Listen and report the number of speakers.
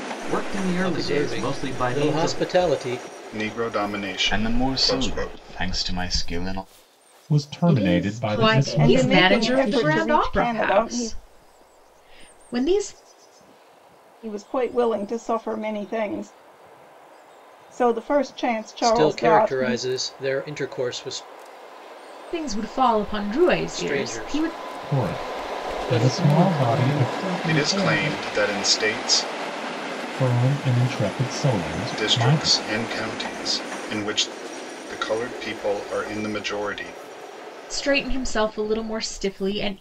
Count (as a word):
eight